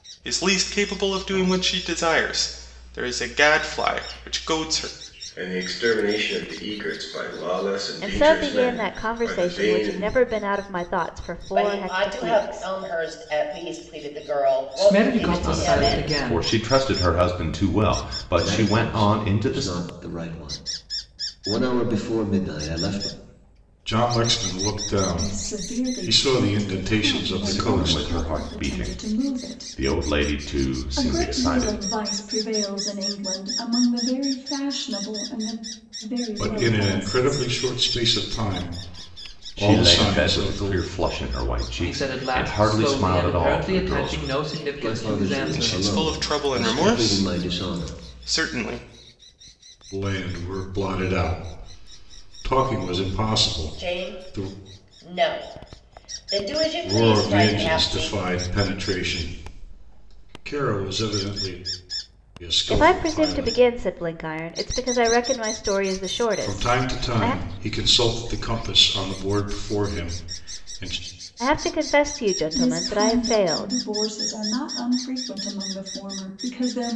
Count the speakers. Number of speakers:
nine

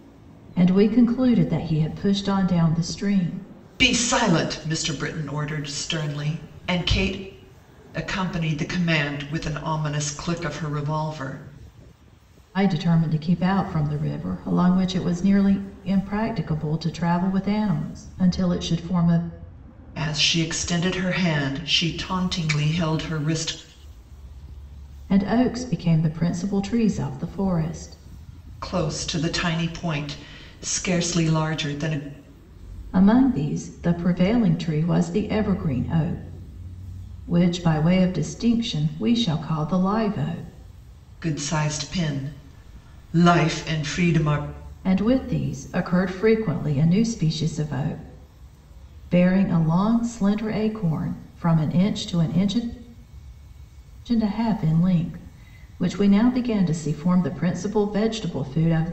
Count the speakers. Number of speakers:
two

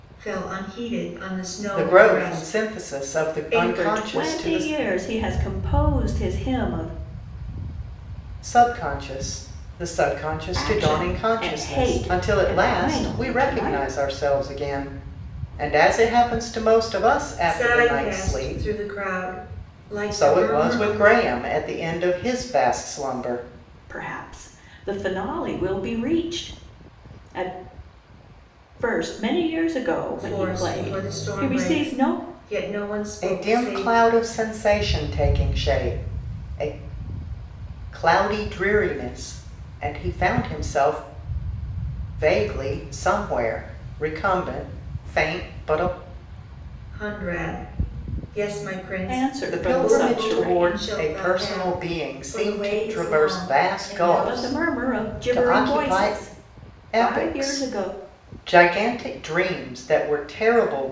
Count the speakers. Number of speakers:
three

